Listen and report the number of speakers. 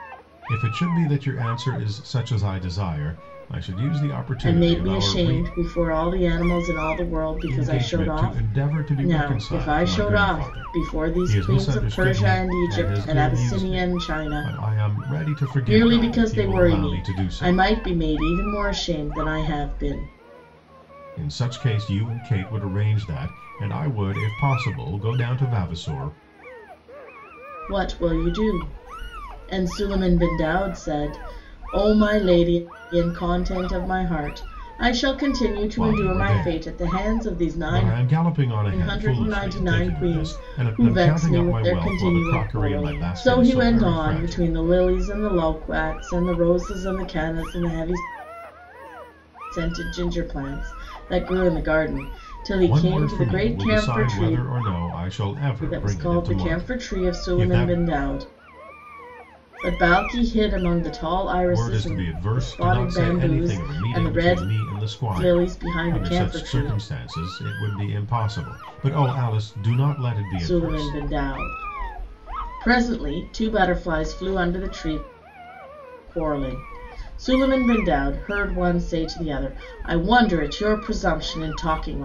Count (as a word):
two